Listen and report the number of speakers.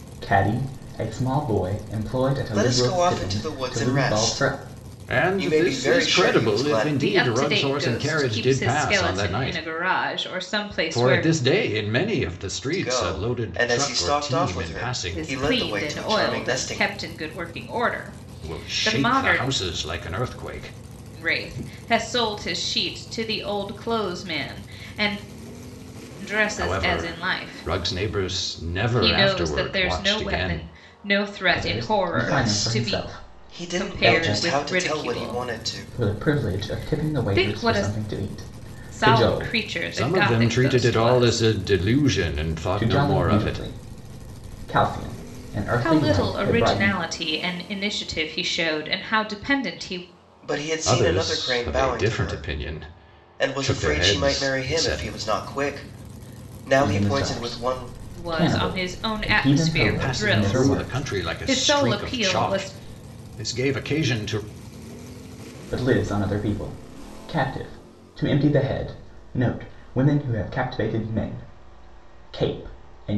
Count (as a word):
four